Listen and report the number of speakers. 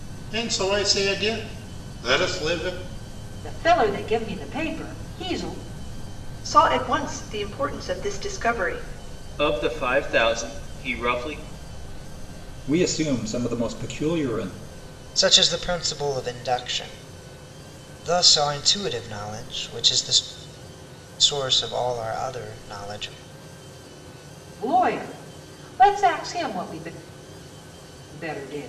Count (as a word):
six